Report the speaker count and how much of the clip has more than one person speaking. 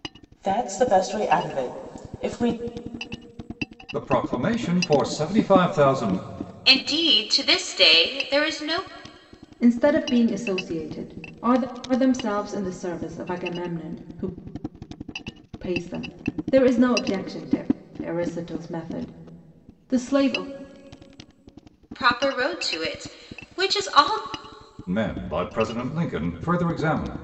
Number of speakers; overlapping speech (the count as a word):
four, no overlap